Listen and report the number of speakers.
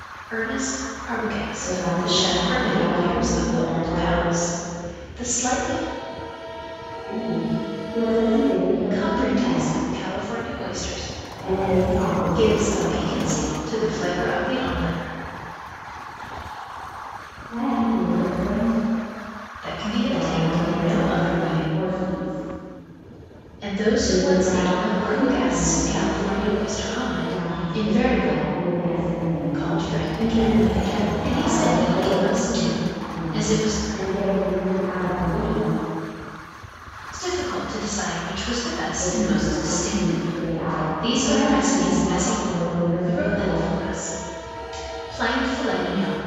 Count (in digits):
2